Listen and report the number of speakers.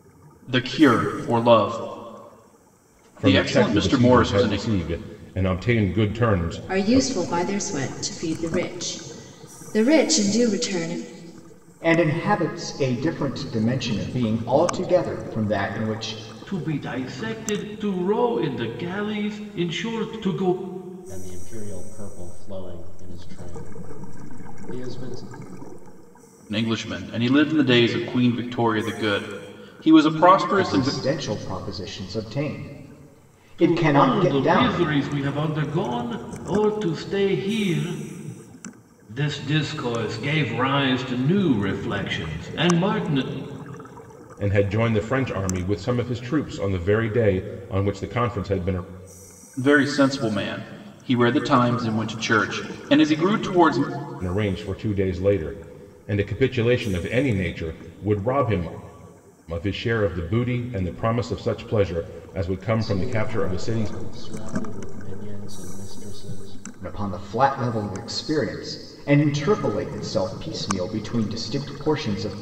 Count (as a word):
six